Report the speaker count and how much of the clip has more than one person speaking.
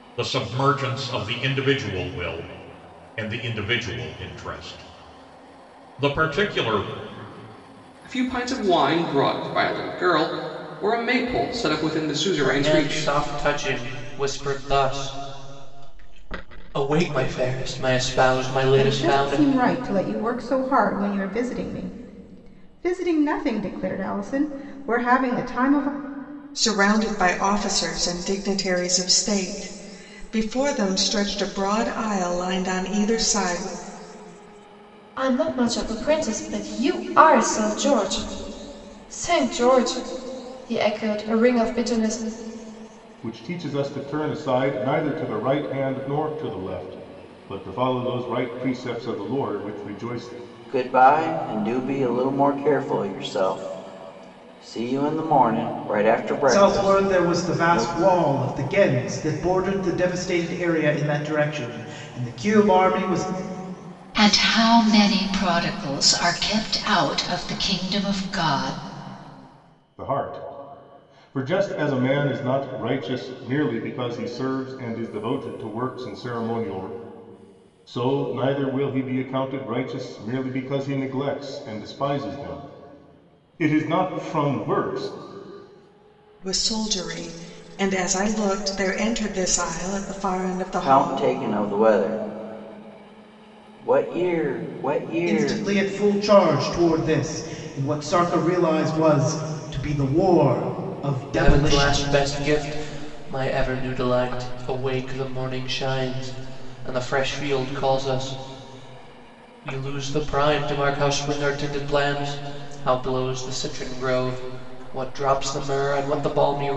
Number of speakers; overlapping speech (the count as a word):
ten, about 4%